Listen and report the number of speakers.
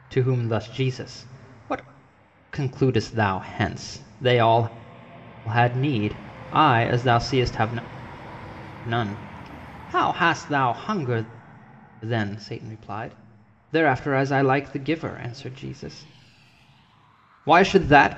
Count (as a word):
one